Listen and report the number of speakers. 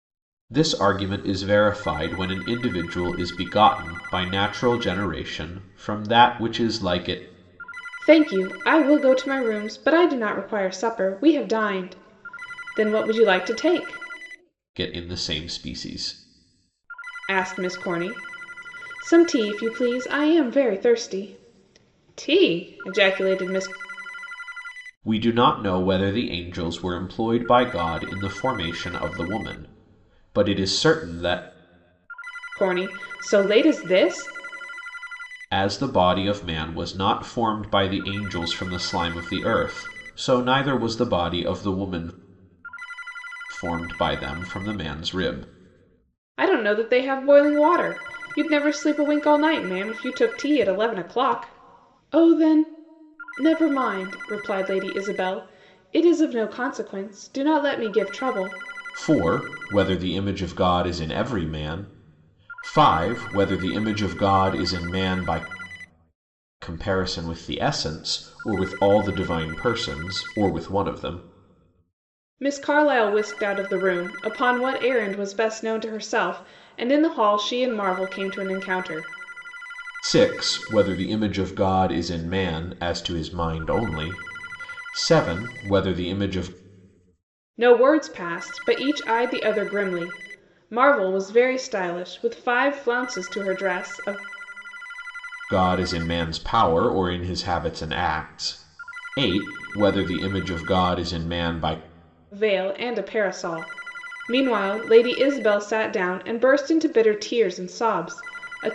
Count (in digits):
2